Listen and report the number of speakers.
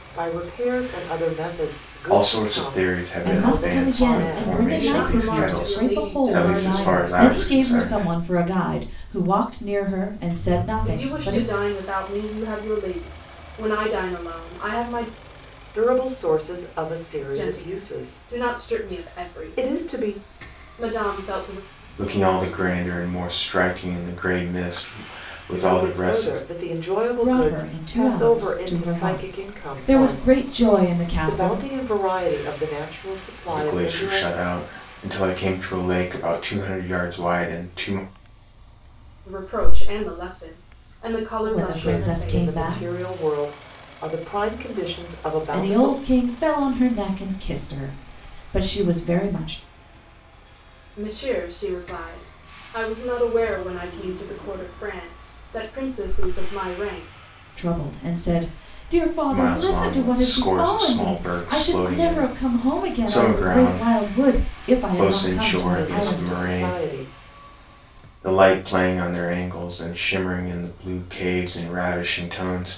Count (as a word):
four